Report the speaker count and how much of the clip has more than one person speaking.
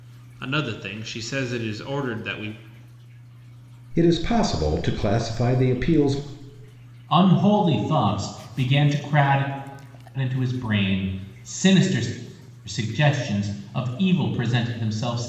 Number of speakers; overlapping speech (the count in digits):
3, no overlap